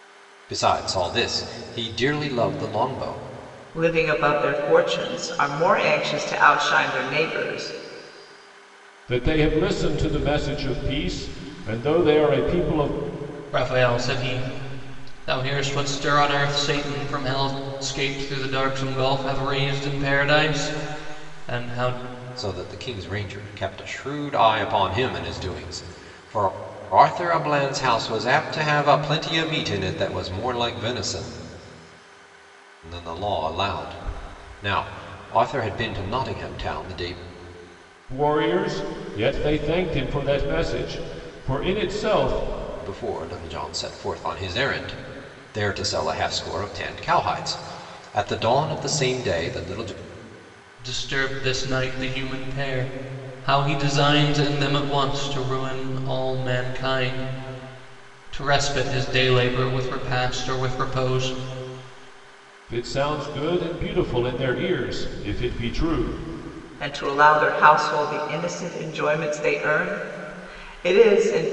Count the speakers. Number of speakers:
four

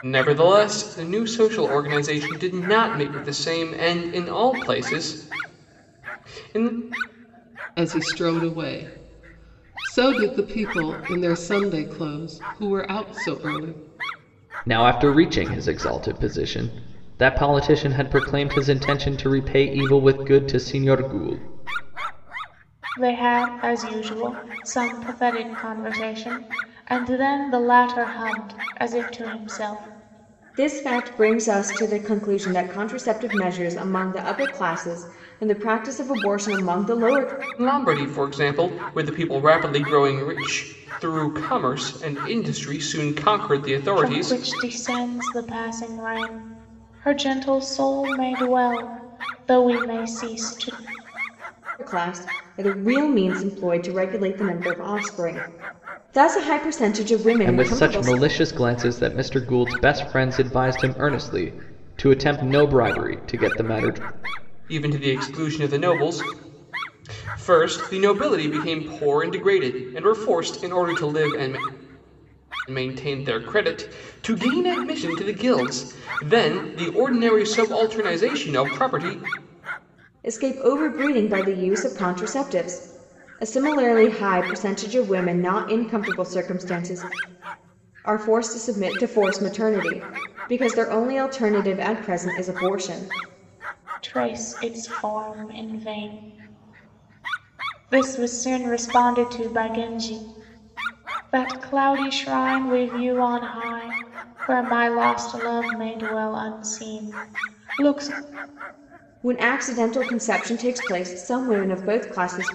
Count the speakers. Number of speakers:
five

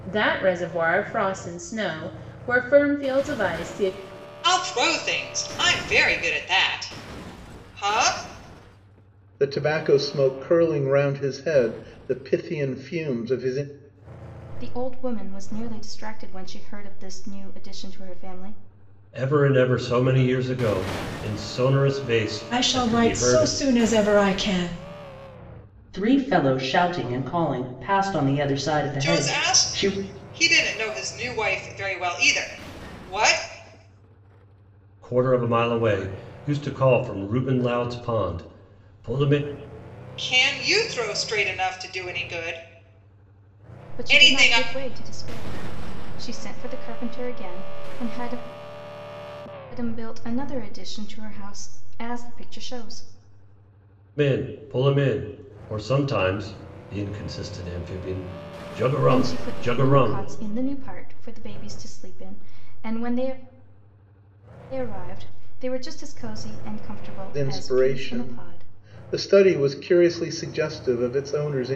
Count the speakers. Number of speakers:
seven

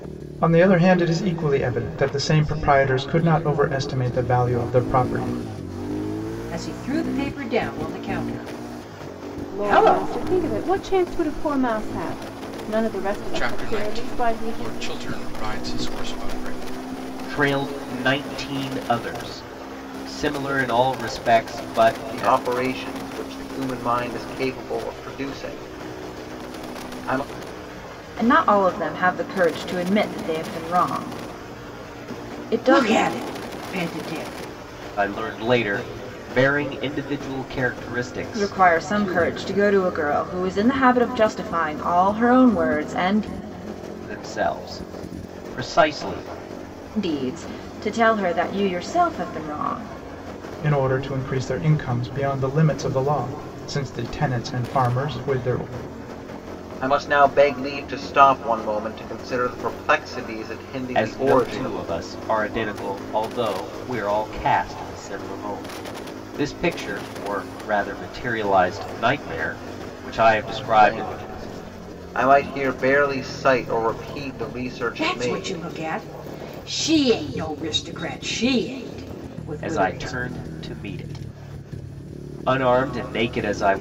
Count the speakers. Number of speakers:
seven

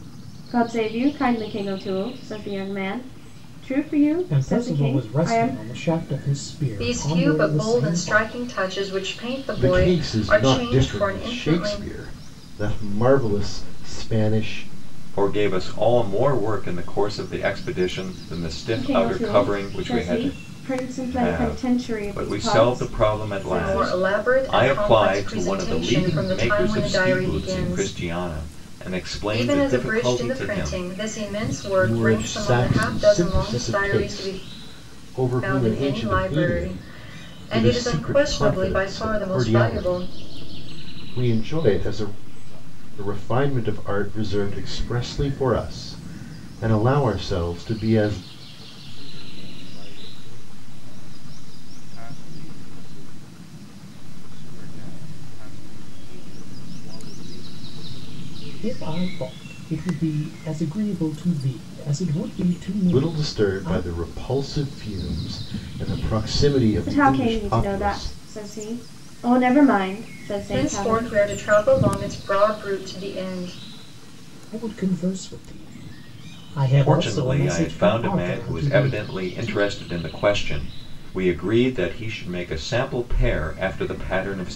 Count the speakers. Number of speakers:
six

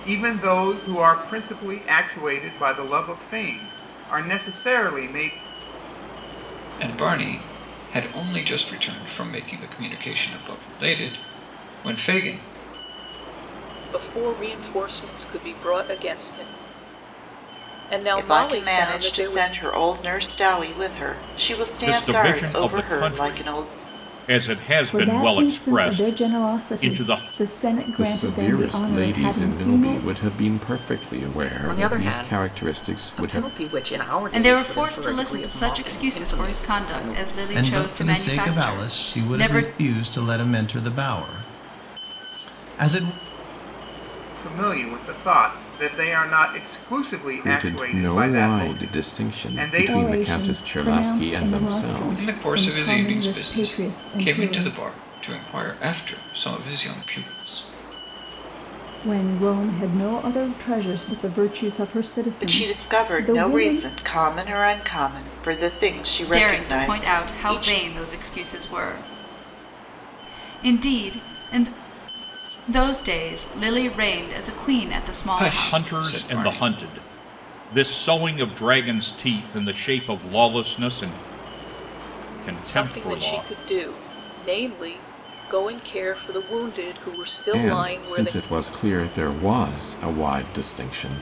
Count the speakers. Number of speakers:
ten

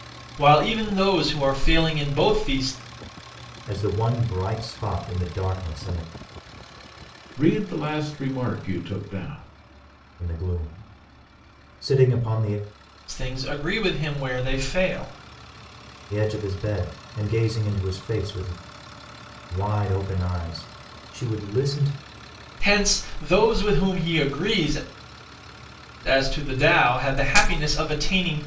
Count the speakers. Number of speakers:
three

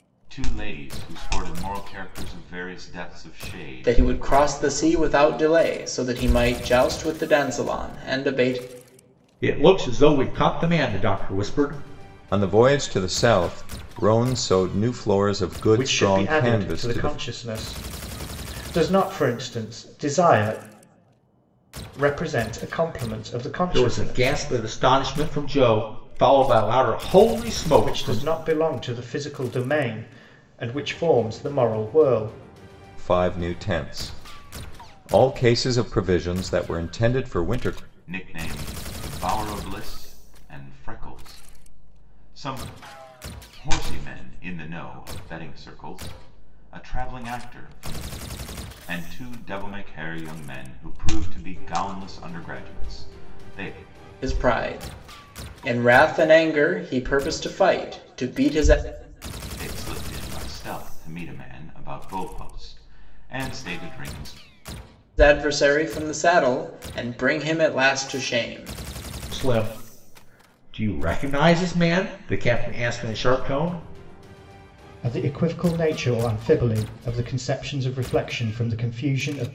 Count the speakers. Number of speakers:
five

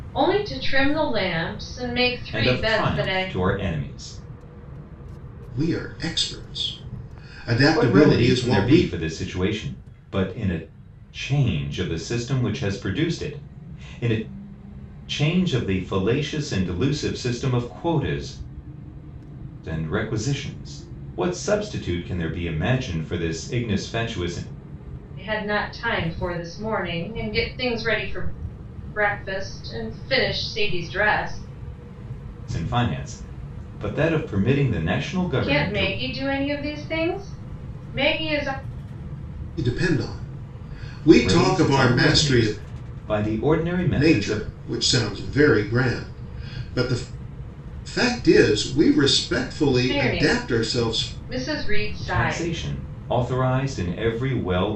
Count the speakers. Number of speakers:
three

